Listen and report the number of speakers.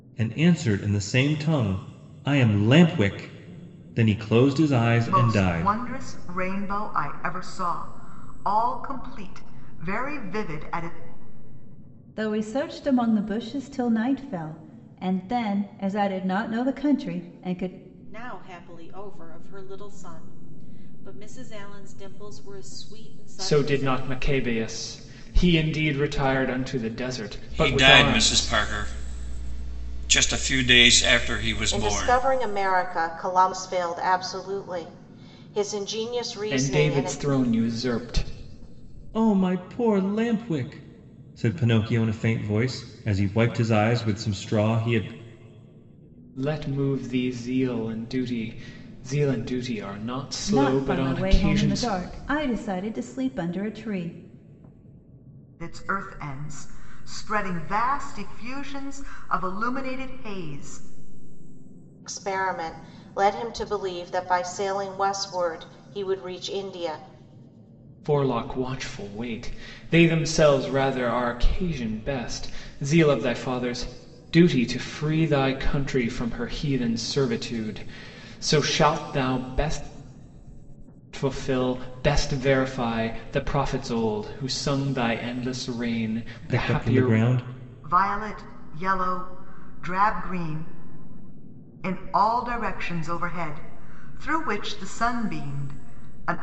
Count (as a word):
seven